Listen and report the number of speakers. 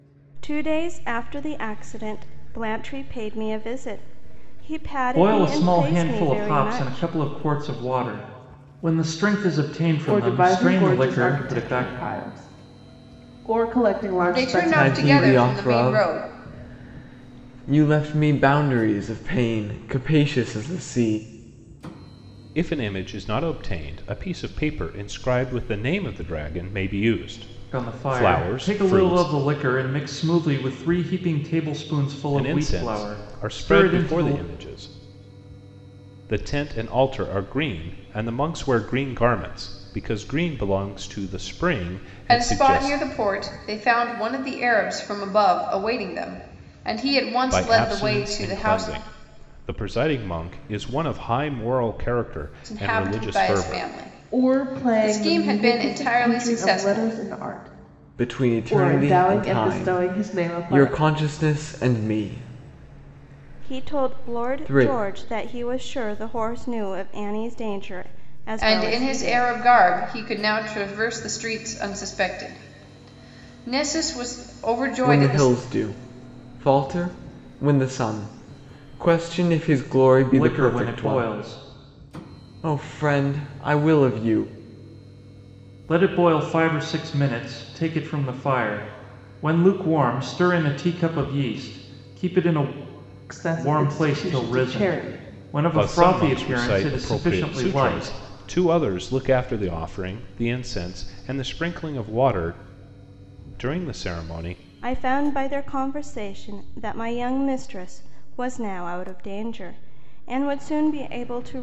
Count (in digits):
6